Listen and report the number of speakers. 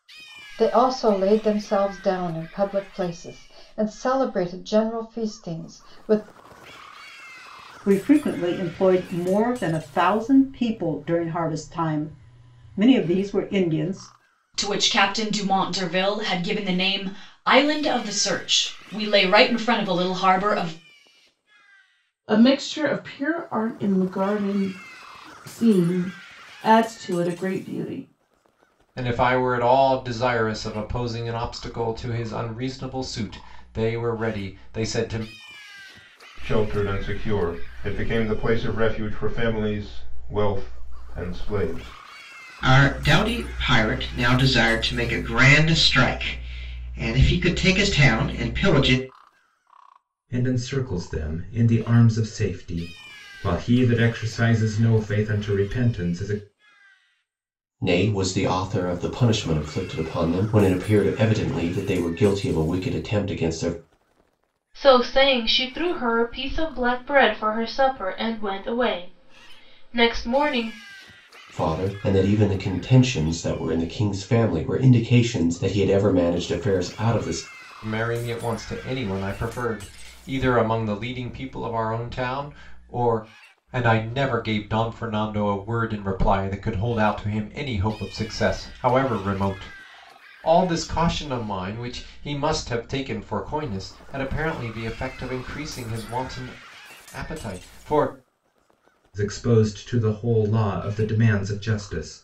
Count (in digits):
10